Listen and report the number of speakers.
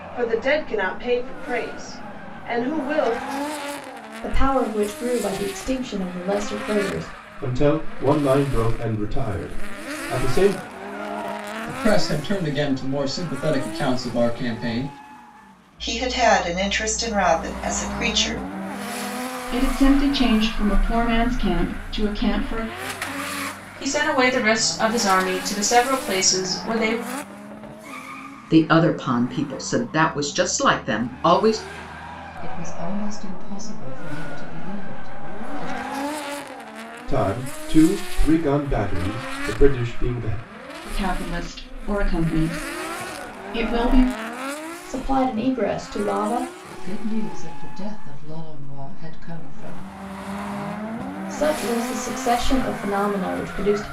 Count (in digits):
9